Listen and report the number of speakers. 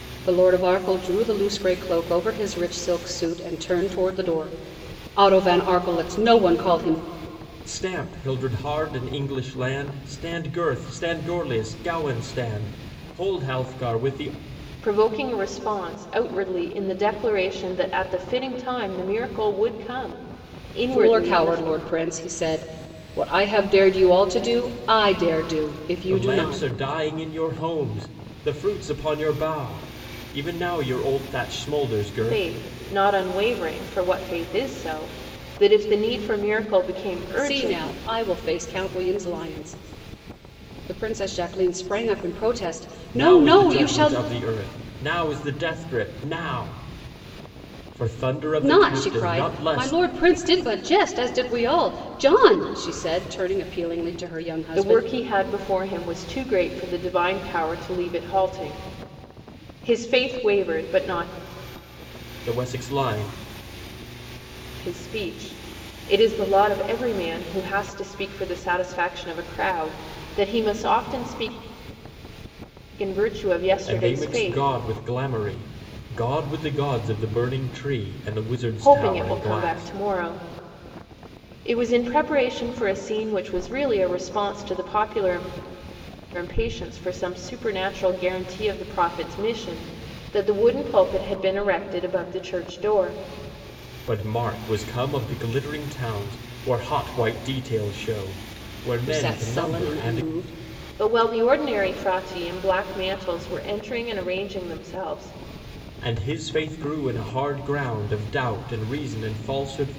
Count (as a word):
three